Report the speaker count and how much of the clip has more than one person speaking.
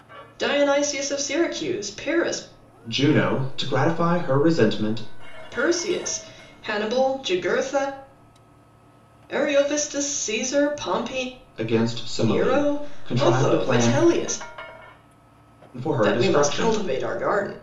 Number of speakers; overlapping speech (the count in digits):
2, about 15%